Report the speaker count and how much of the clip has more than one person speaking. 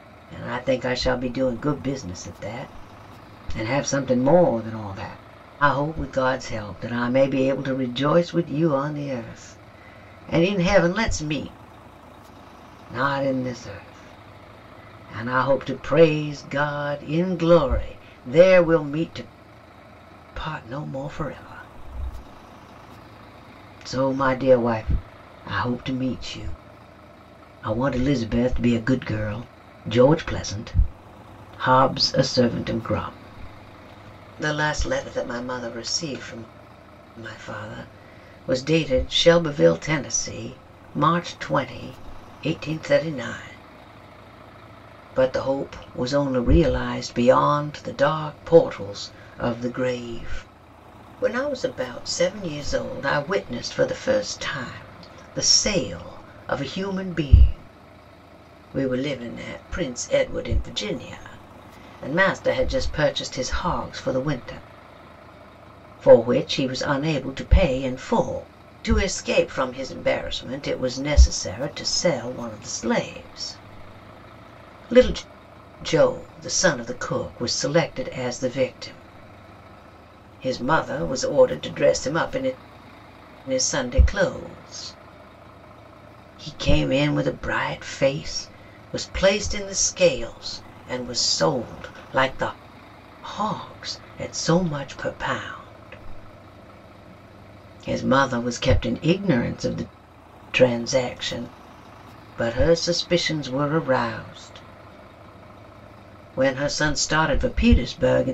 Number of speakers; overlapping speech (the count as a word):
one, no overlap